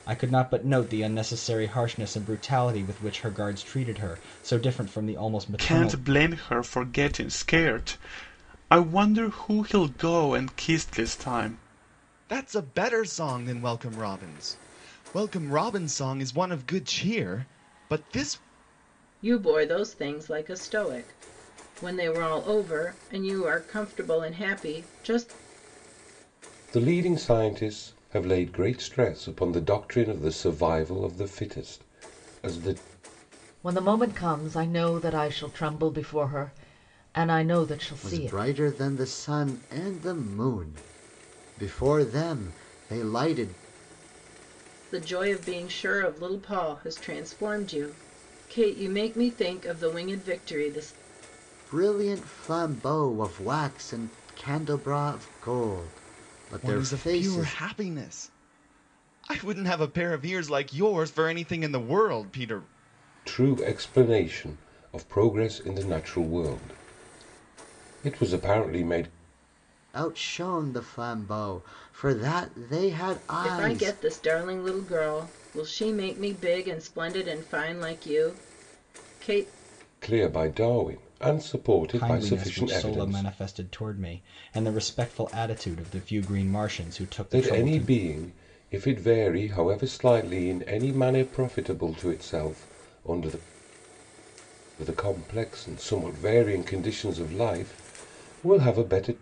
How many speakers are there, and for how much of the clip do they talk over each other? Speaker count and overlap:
seven, about 5%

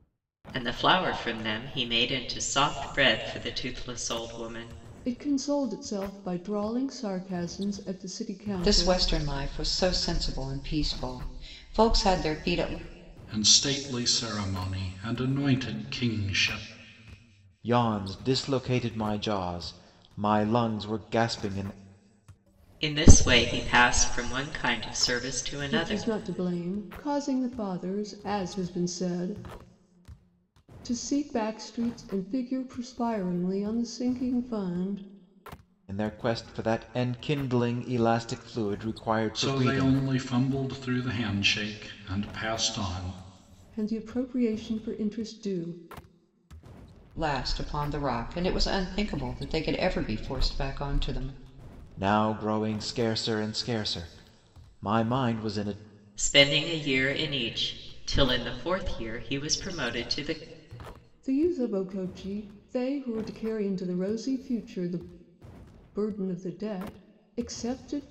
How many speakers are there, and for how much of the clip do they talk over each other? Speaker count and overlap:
five, about 2%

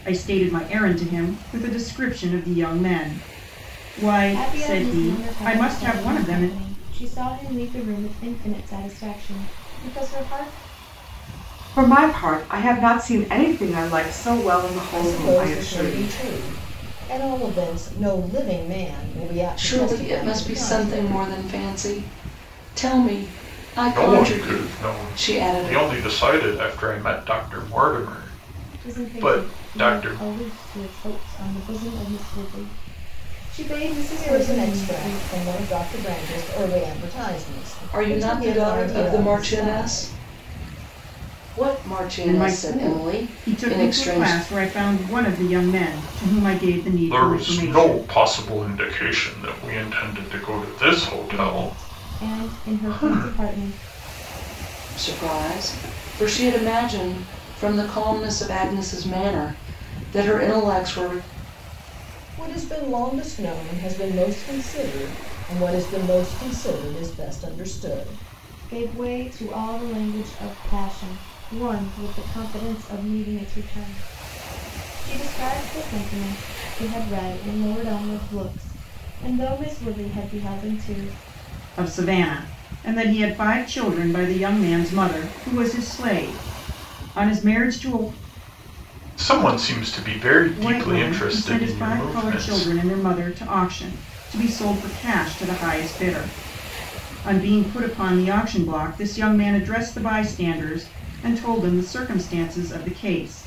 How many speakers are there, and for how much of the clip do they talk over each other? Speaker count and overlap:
six, about 19%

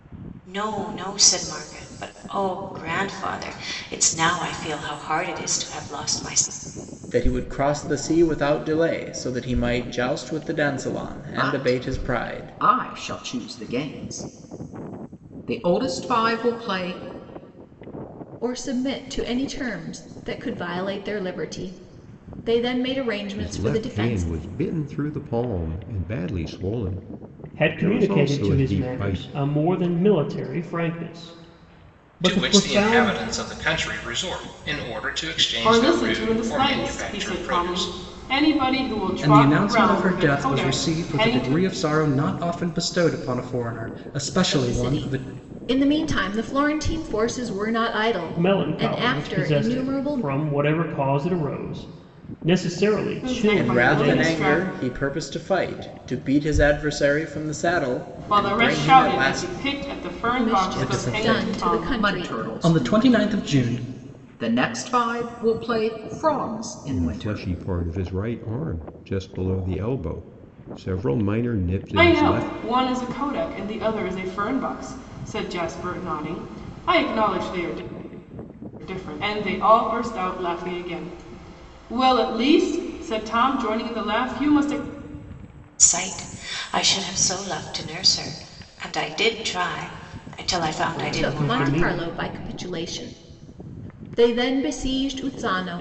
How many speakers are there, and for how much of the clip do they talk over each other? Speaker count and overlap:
nine, about 22%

